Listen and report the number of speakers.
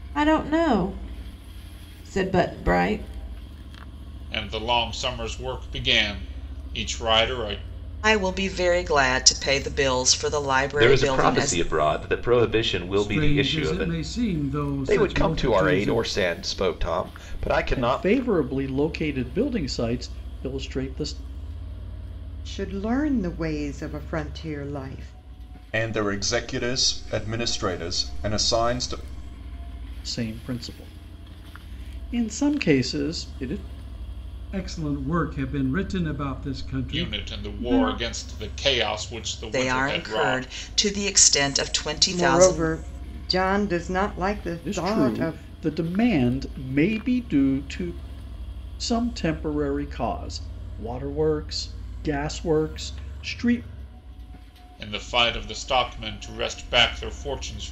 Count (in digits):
9